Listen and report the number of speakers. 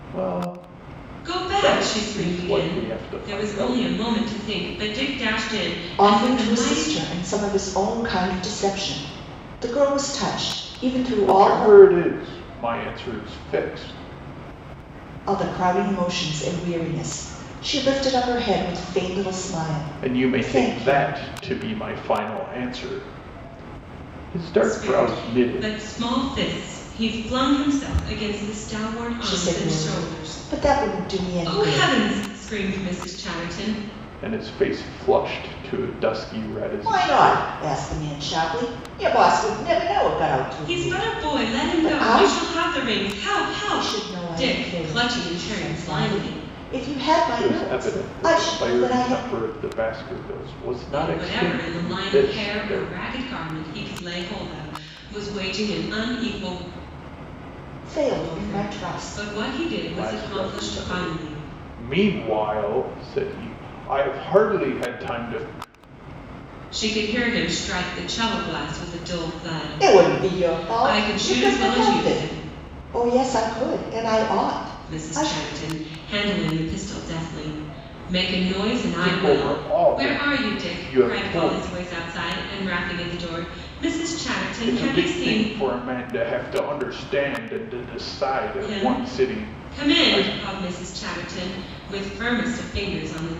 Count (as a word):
three